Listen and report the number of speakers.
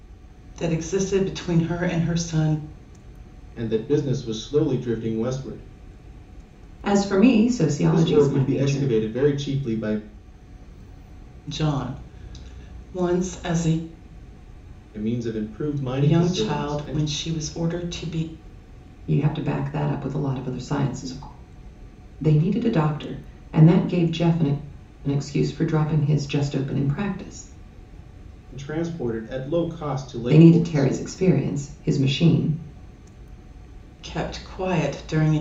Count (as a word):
three